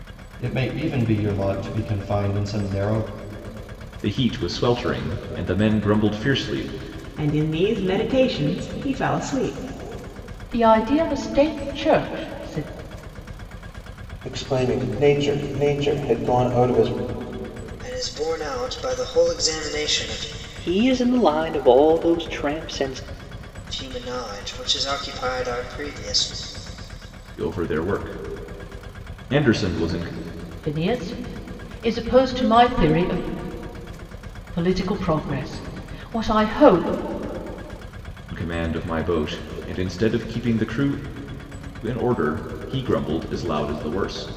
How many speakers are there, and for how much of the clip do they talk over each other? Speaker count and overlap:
7, no overlap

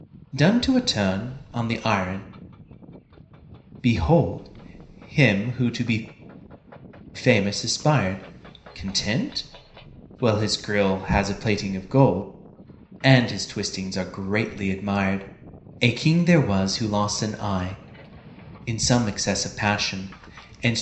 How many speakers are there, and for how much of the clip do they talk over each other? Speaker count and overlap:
1, no overlap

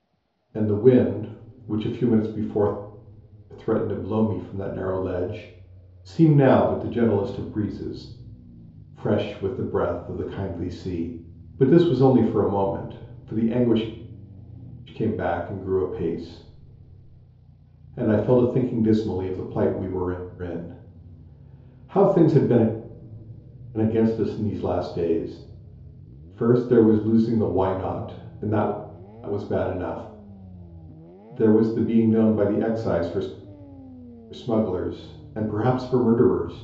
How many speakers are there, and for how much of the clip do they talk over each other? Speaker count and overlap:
1, no overlap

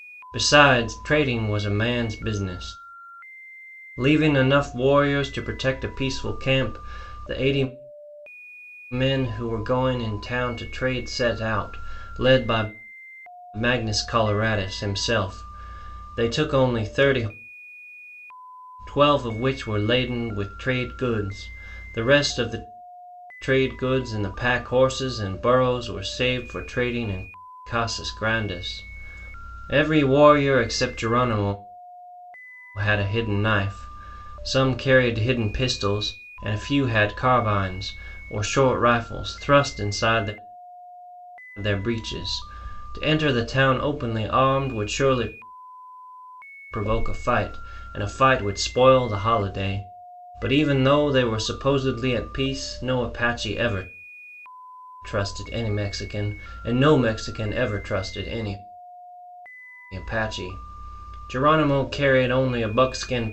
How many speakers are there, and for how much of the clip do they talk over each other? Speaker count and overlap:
1, no overlap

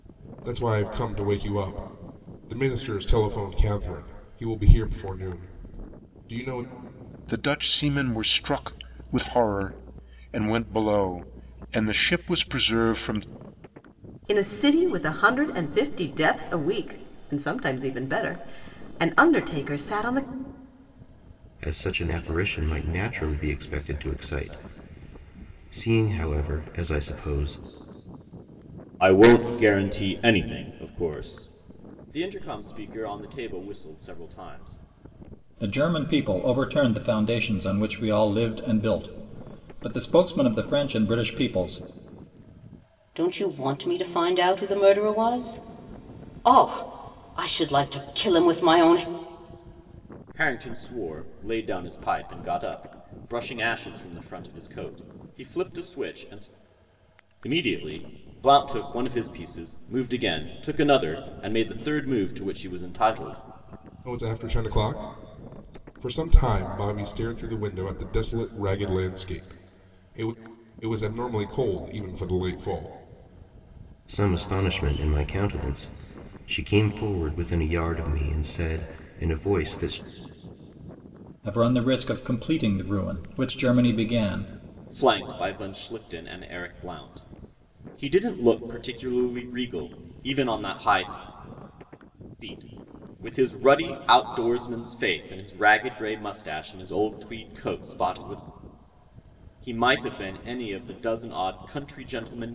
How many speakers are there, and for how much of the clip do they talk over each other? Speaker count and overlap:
7, no overlap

